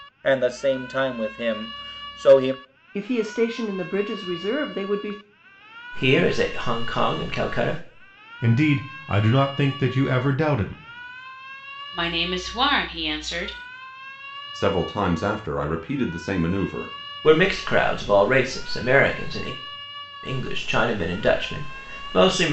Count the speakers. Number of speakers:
6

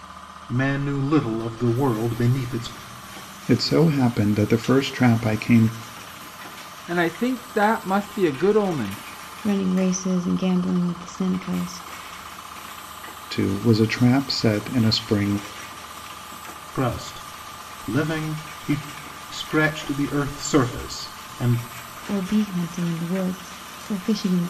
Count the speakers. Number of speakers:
4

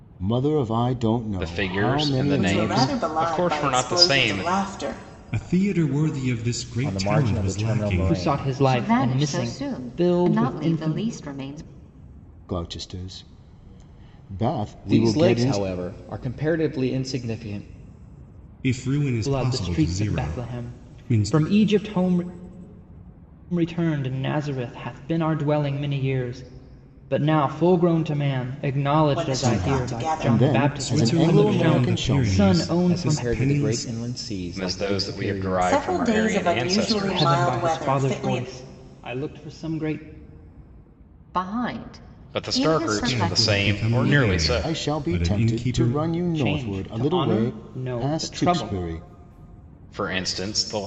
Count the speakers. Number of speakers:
7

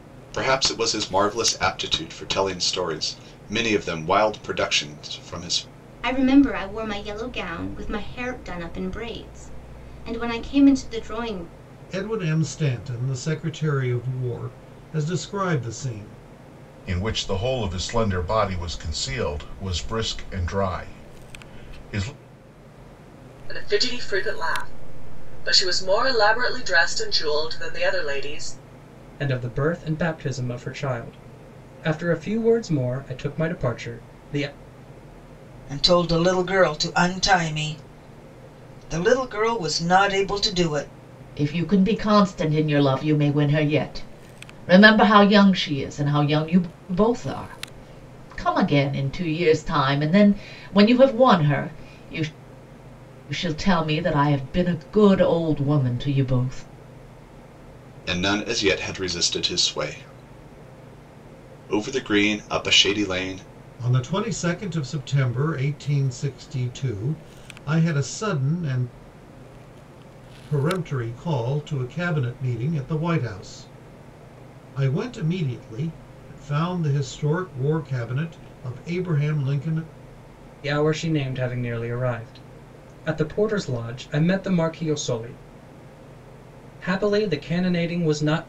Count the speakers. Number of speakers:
8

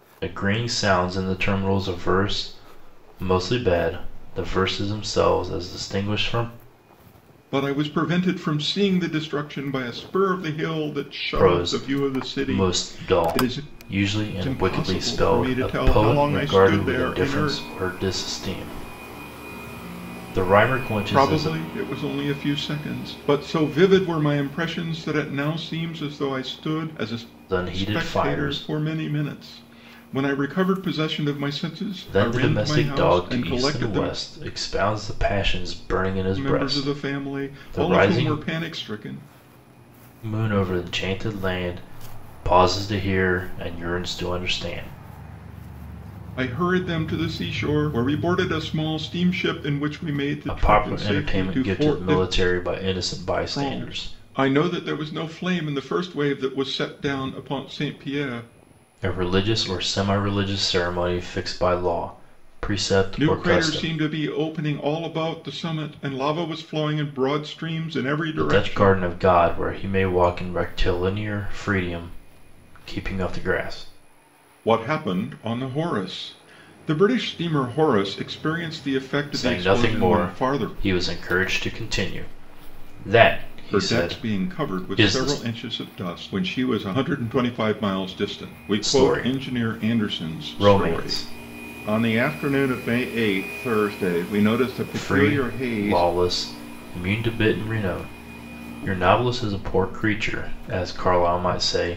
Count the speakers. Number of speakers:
2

